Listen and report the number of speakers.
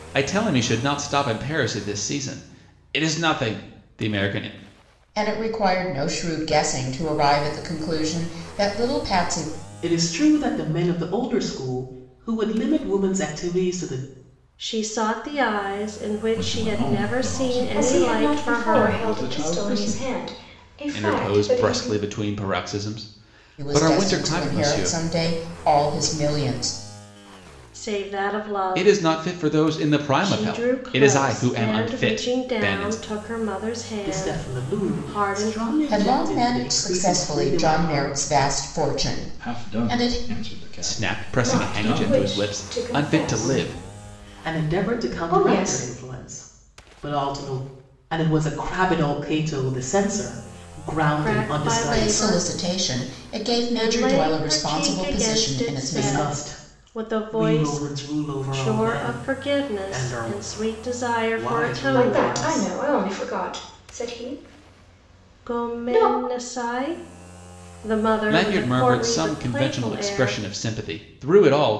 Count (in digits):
6